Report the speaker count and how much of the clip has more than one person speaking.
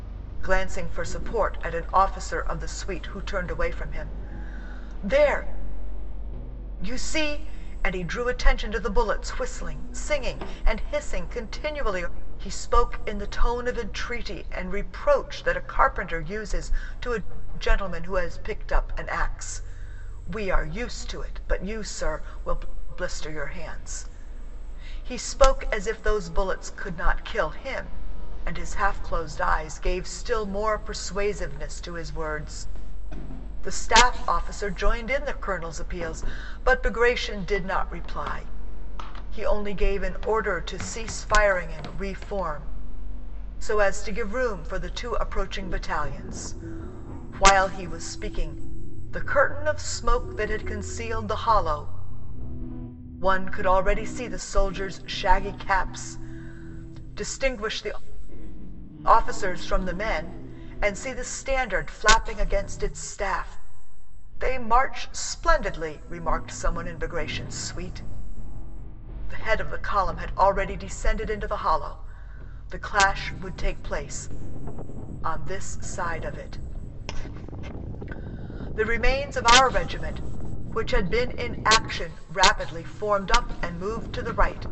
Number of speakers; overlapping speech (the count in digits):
1, no overlap